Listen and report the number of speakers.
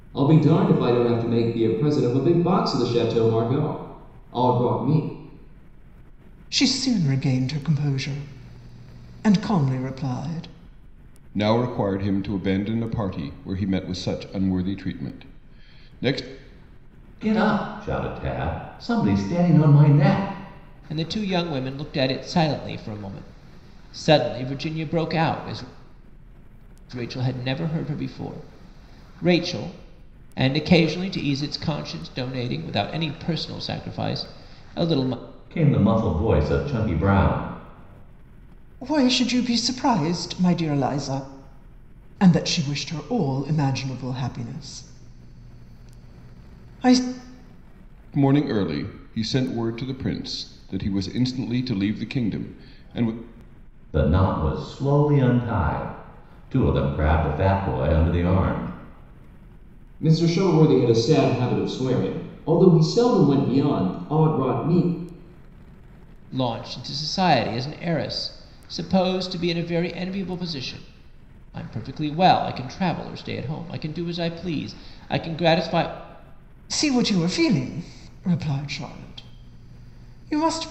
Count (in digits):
5